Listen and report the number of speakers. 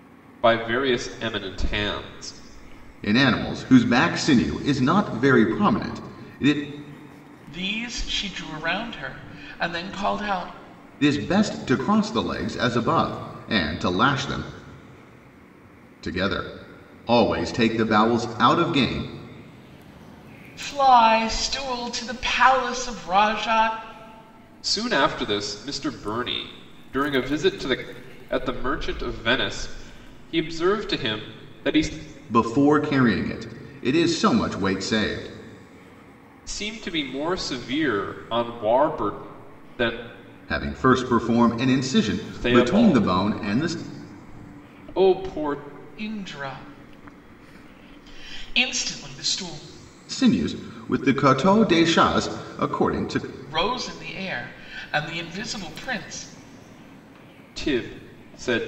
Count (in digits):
3